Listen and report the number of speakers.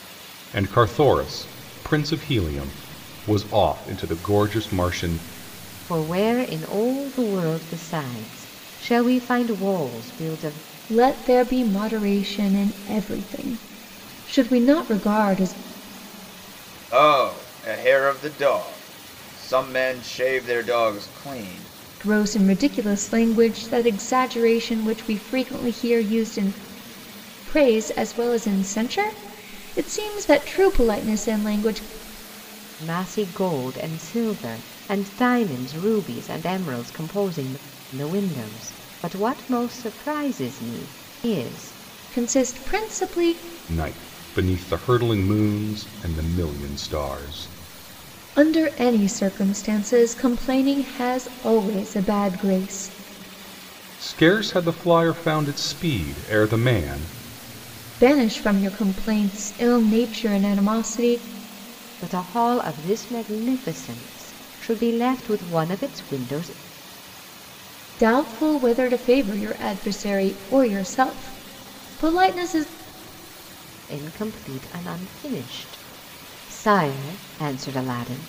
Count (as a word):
four